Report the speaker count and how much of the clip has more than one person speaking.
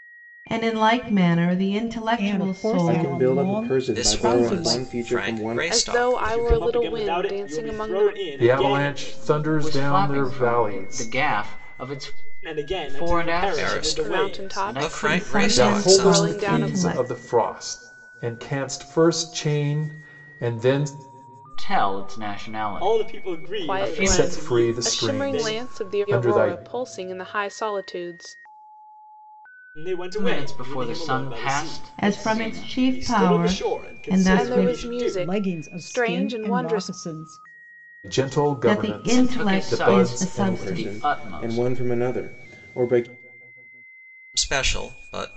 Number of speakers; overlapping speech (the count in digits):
9, about 60%